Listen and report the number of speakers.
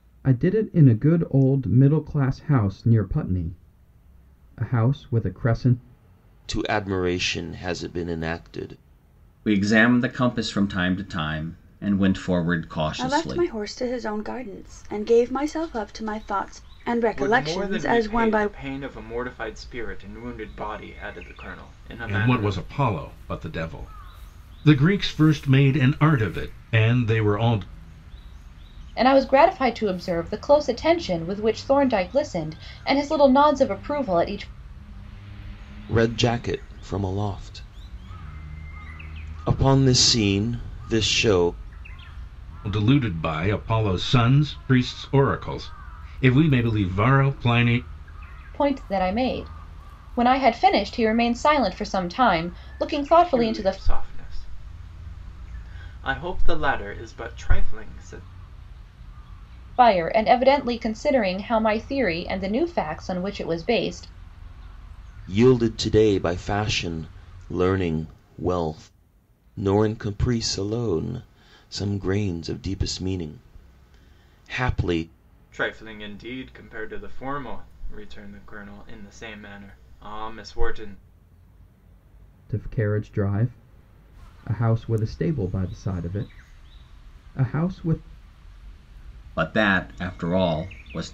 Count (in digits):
7